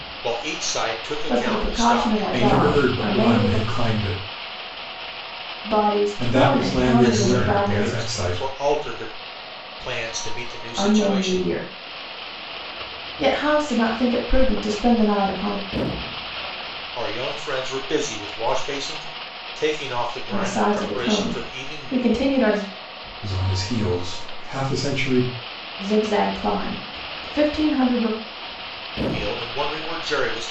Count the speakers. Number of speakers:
3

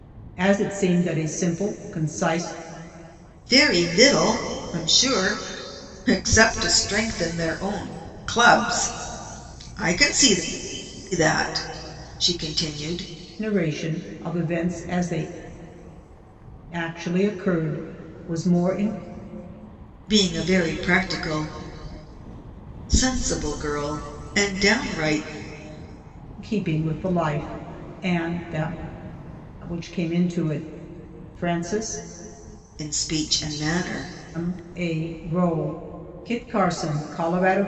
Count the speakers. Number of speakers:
2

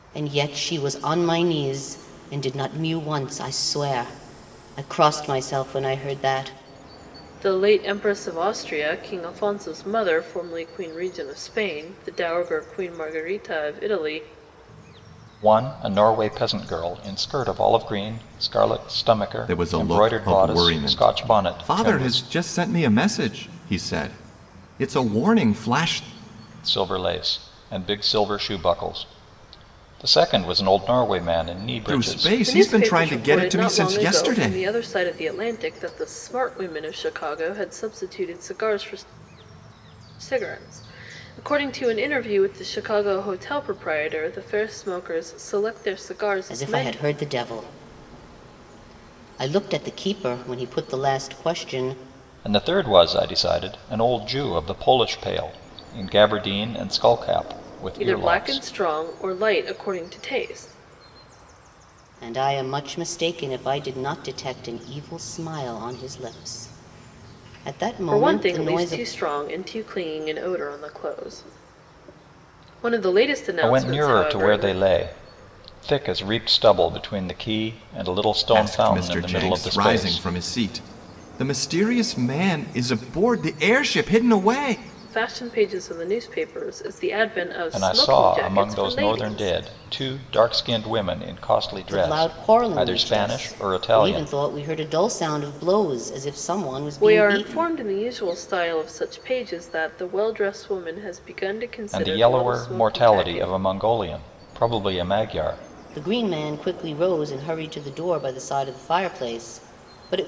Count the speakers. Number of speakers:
4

